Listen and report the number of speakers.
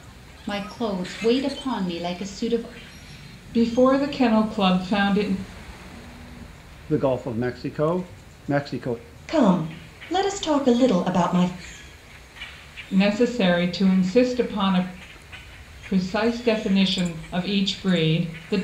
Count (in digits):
4